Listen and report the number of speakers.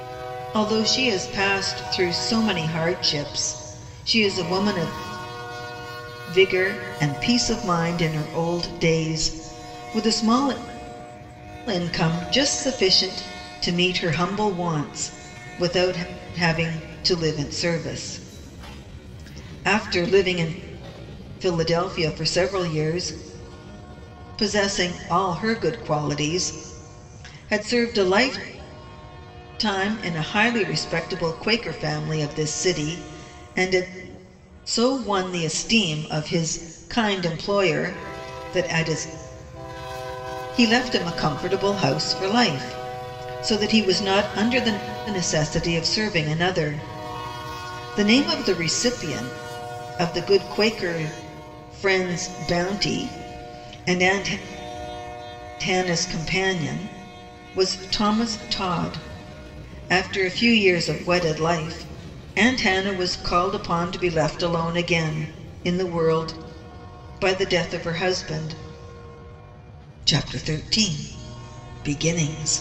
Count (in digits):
1